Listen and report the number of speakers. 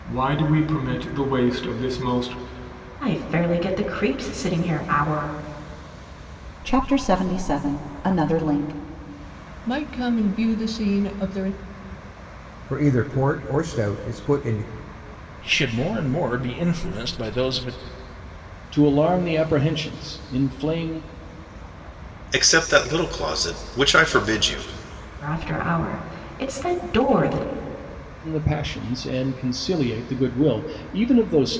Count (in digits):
8